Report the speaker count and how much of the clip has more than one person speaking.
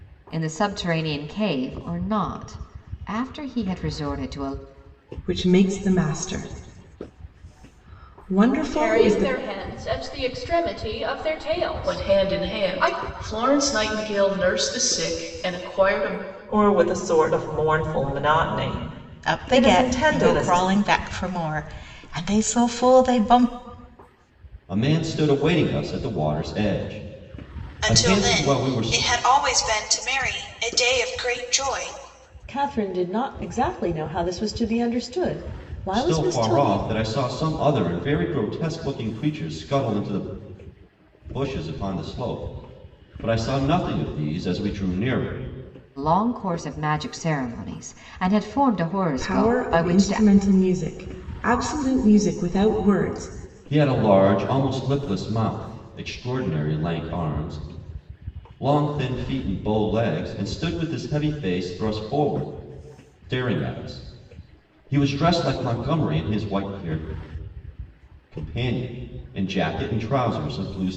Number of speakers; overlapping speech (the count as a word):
nine, about 9%